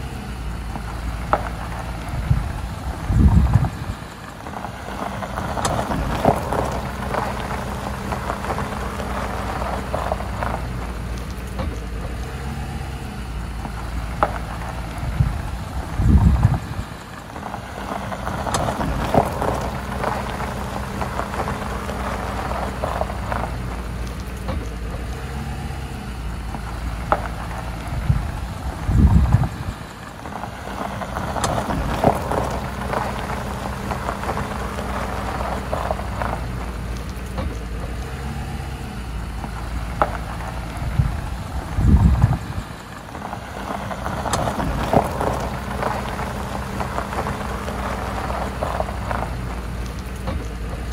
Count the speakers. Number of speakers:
zero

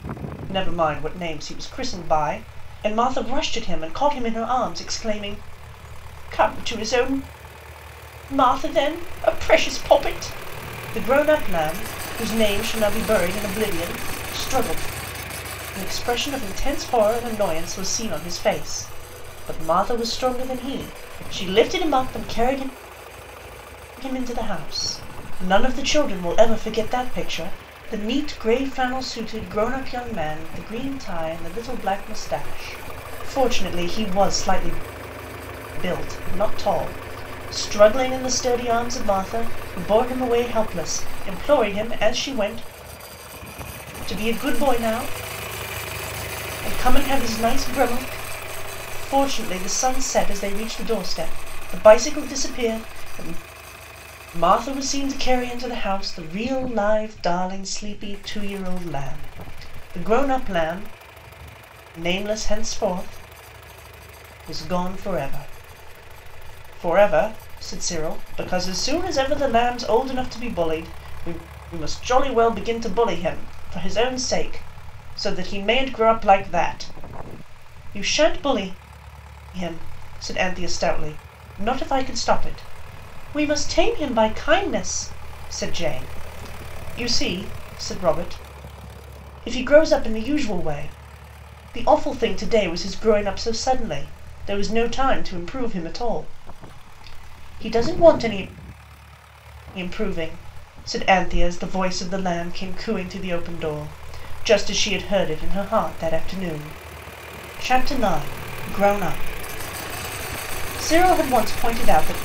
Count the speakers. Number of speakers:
one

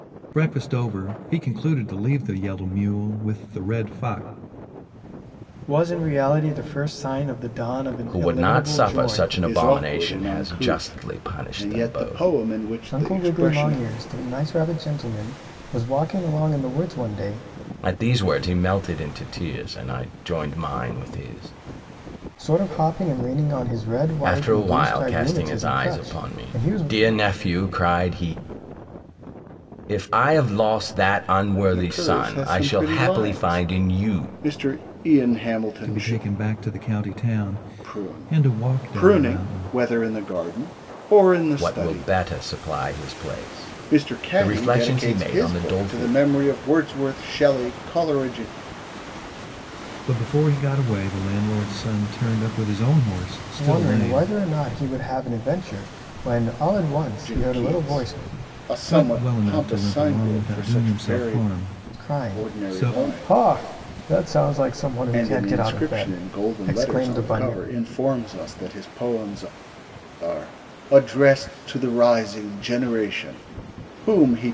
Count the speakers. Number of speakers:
four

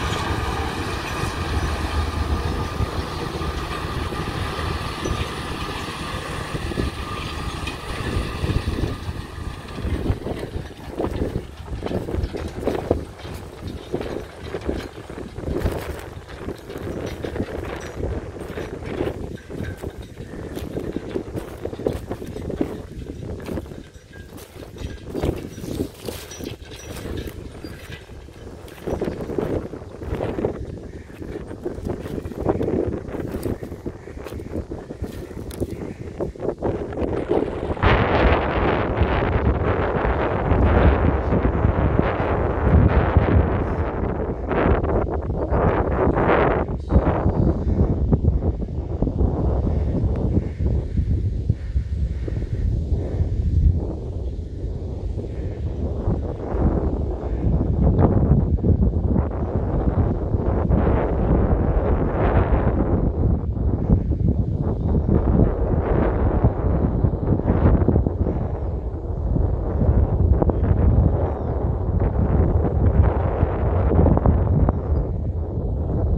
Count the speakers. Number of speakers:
zero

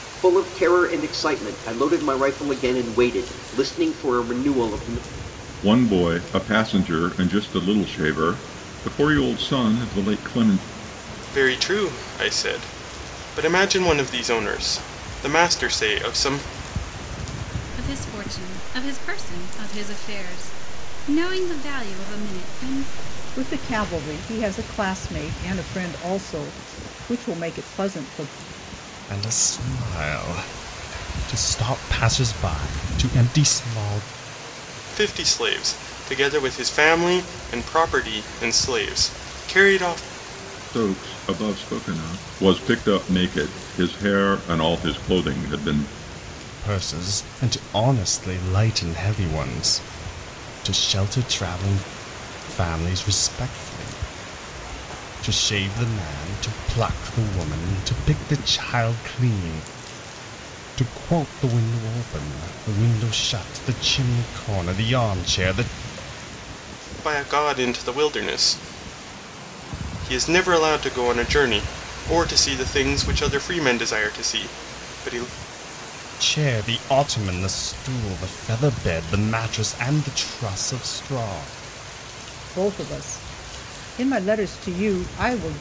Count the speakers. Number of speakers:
six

